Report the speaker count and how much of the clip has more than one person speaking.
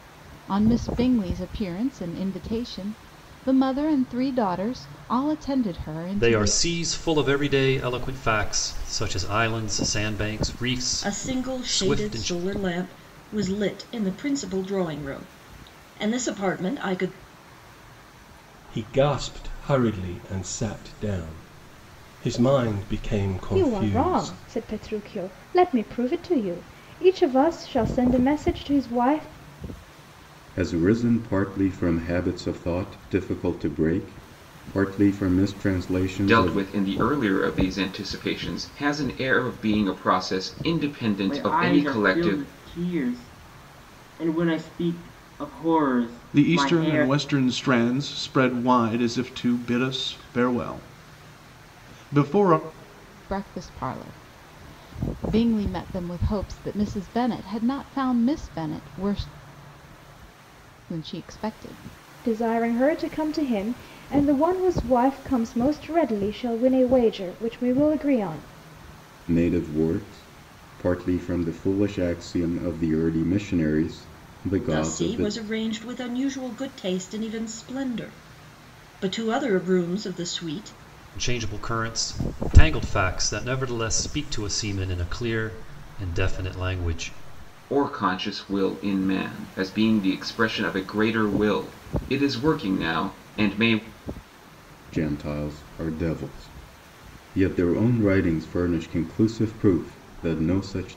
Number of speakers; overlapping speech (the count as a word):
nine, about 6%